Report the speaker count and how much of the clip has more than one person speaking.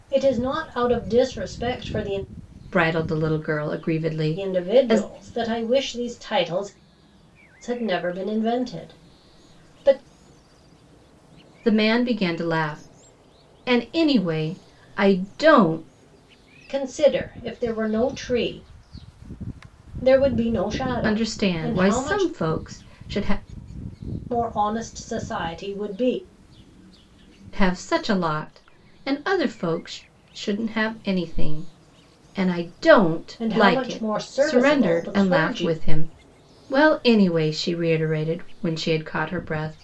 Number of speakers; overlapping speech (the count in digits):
2, about 11%